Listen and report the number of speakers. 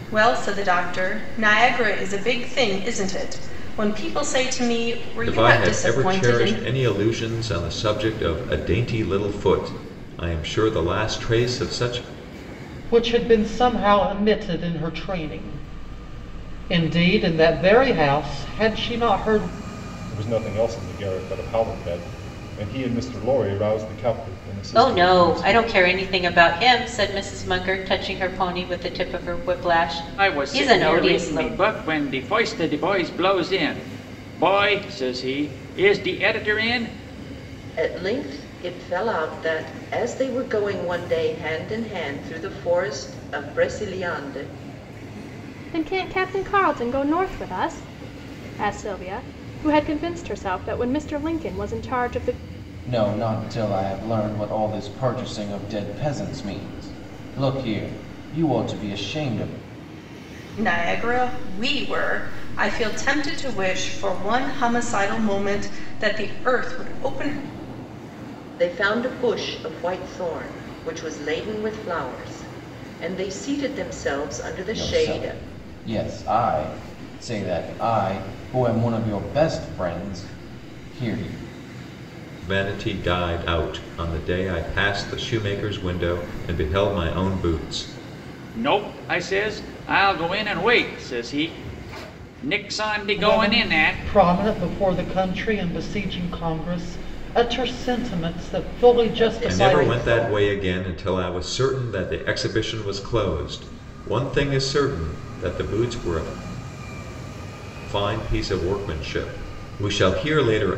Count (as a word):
nine